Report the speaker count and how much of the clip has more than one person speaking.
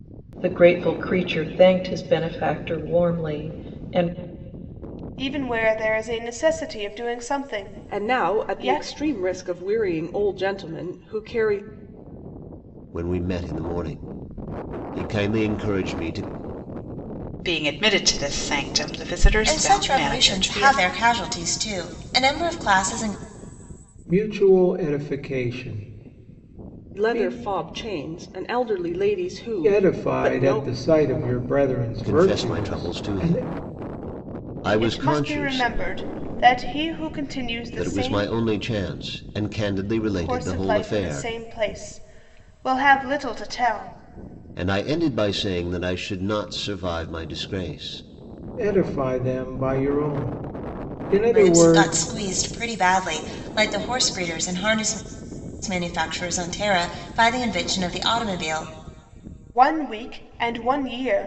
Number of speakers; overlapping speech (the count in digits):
7, about 14%